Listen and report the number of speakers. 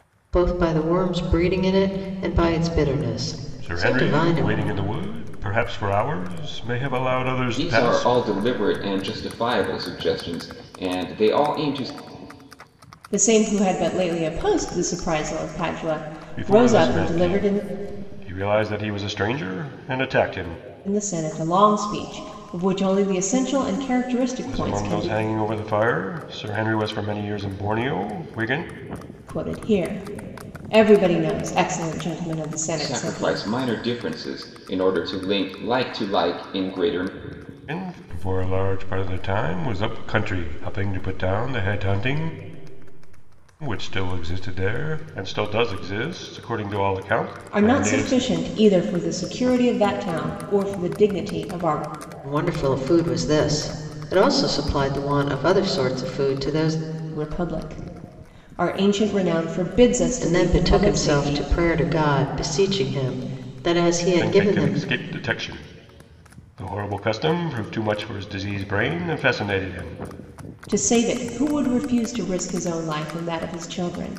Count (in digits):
4